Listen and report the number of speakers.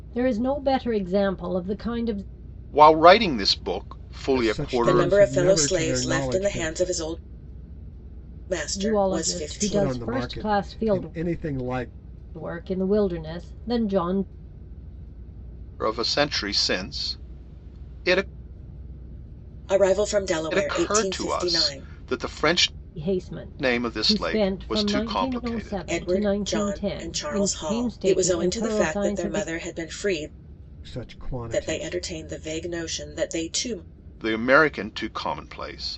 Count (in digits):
4